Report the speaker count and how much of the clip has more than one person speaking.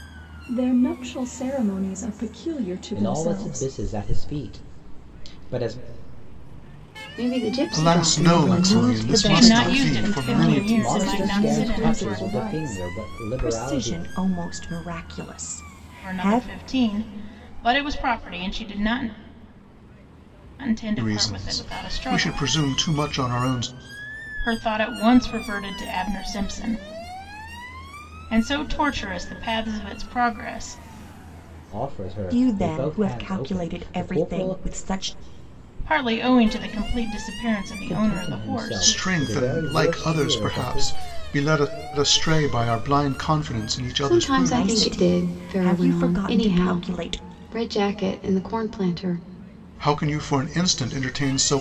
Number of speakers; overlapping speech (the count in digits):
6, about 34%